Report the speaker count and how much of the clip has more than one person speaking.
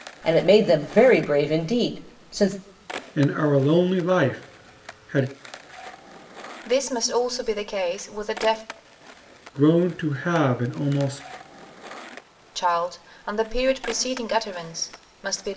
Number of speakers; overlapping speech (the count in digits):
3, no overlap